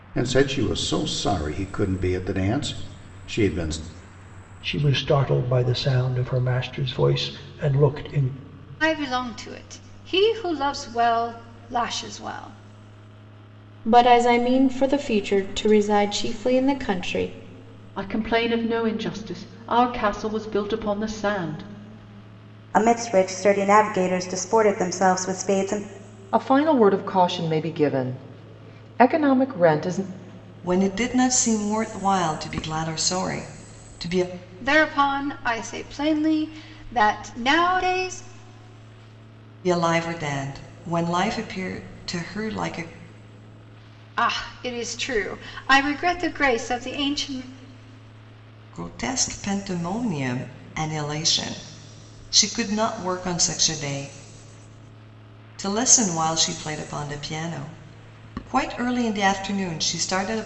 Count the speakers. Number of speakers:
8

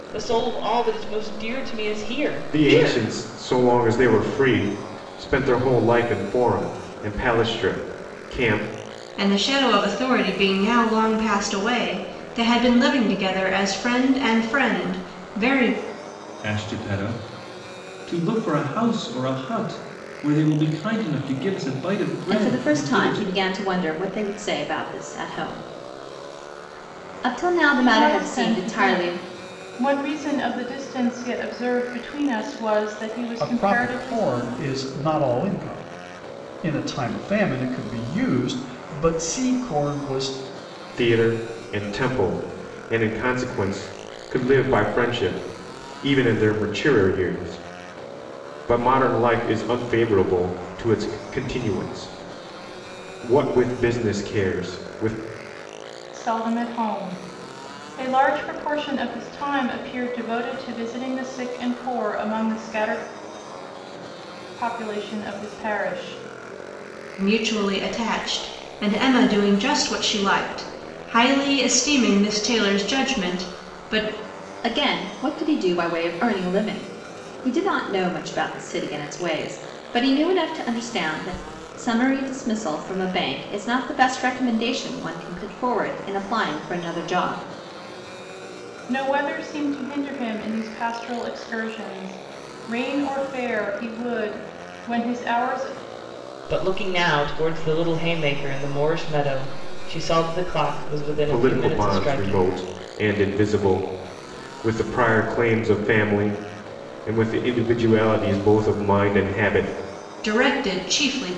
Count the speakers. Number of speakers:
7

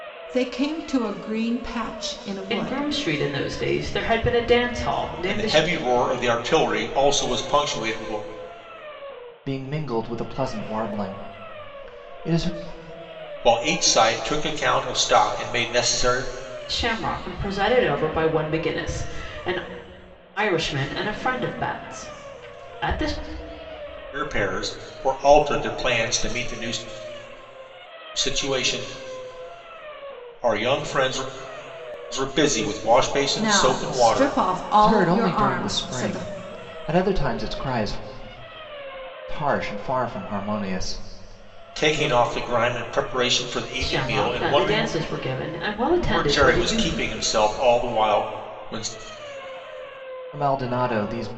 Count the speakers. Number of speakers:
4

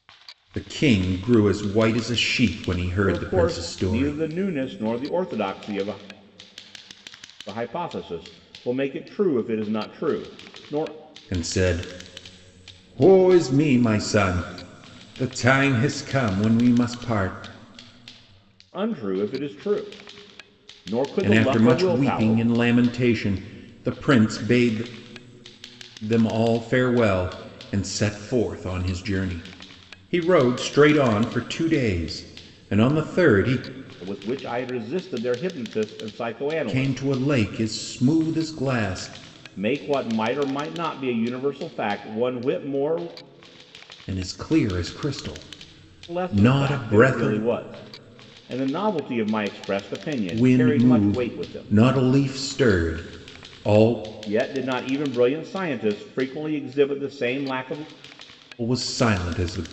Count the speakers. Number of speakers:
2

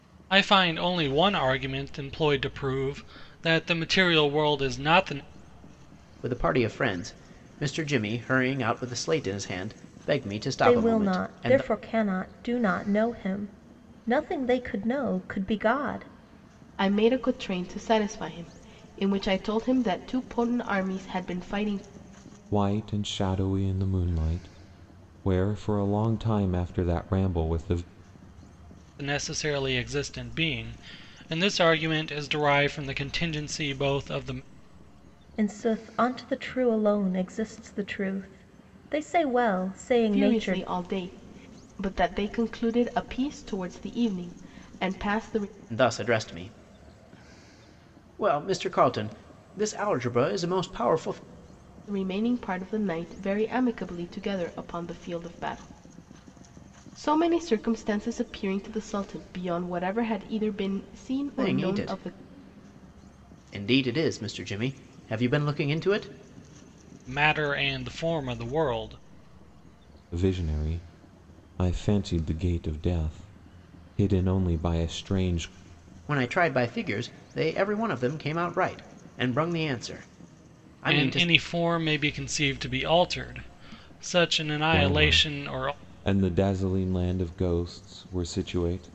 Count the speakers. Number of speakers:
5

